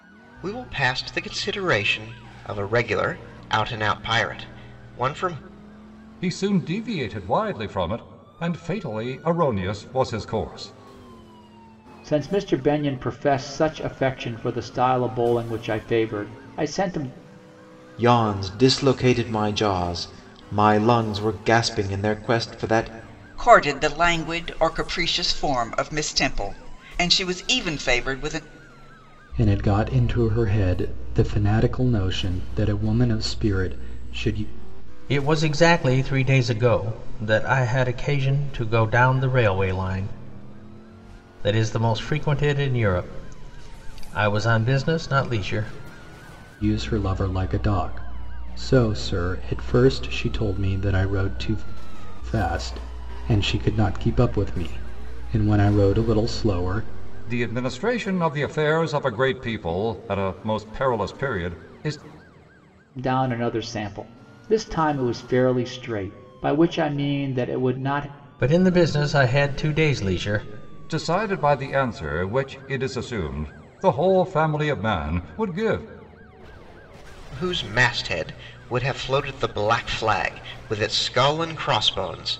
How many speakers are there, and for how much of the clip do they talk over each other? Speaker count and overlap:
7, no overlap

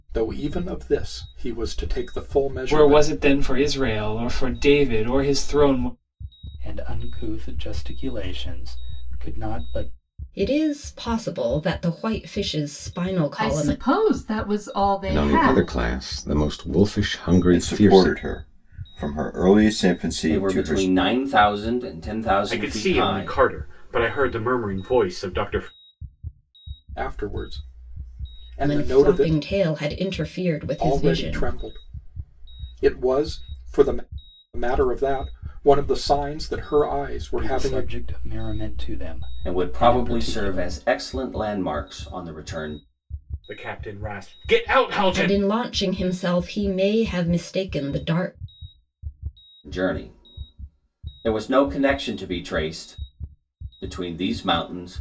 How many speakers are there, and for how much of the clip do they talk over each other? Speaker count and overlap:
9, about 14%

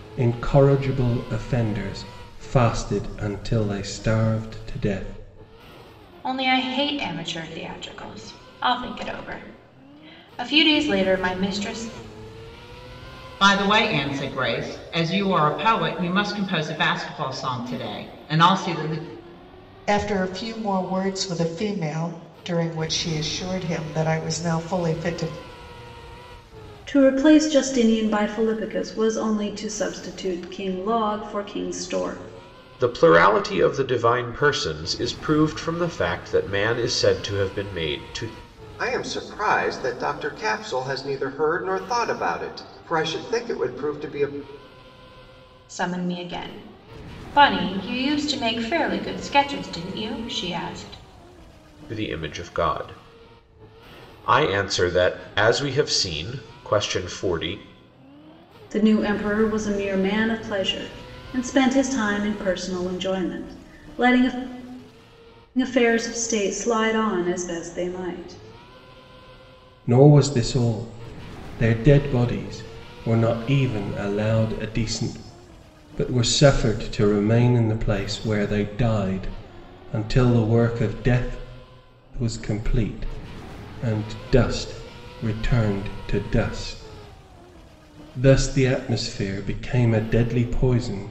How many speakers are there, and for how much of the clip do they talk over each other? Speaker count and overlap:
7, no overlap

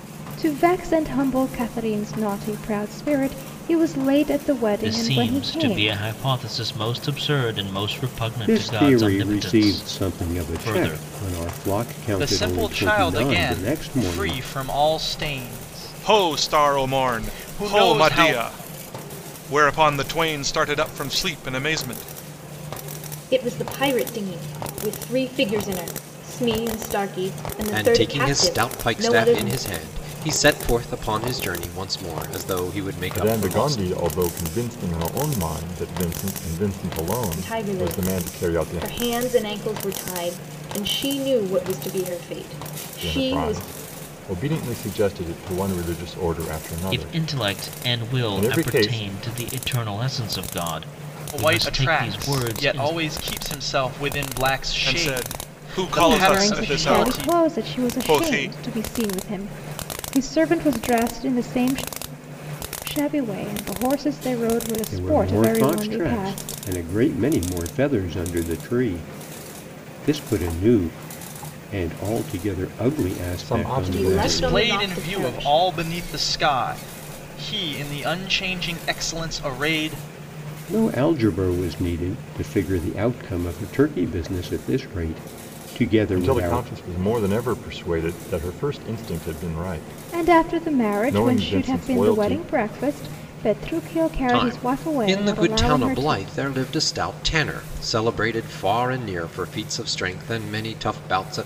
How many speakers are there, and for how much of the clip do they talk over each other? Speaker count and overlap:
8, about 29%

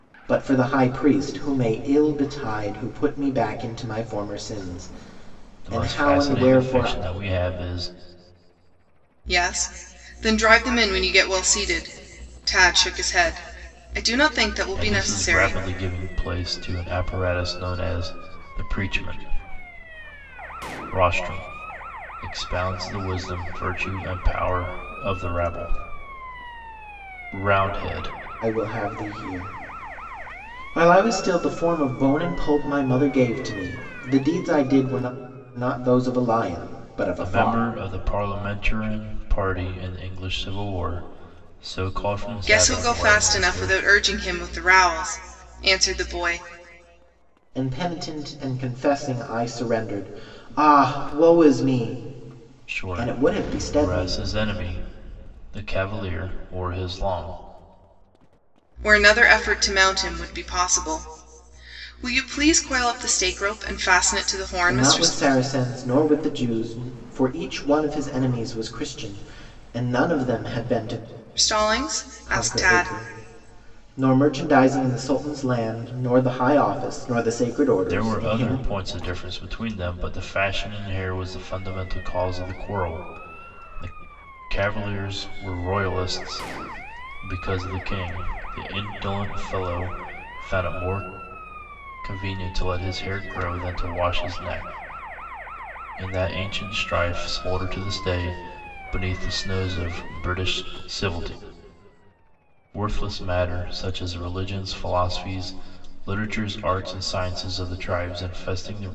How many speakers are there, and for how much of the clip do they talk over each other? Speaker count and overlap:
3, about 7%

